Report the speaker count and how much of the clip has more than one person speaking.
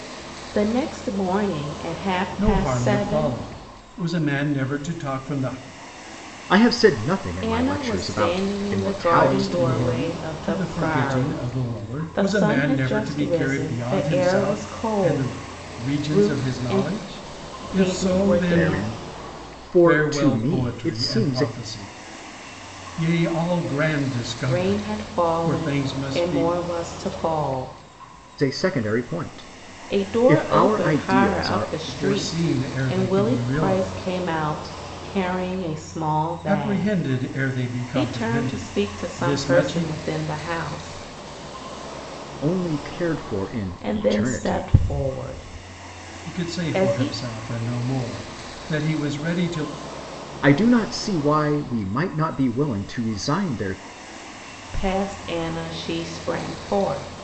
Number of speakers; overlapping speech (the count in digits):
3, about 42%